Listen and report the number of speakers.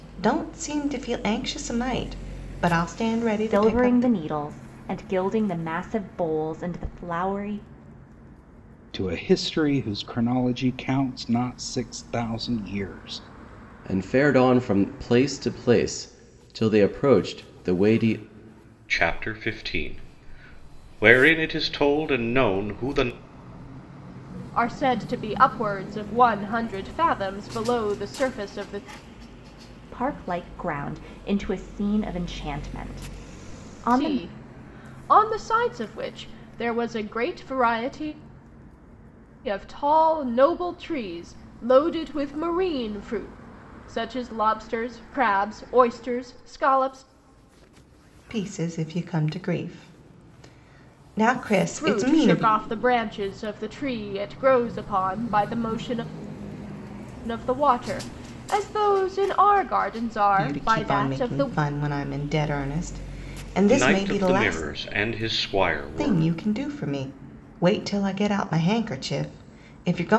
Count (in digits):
6